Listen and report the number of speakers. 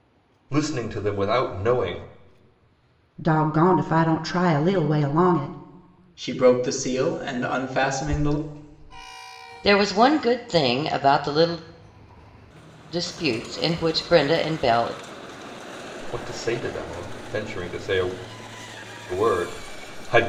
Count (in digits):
4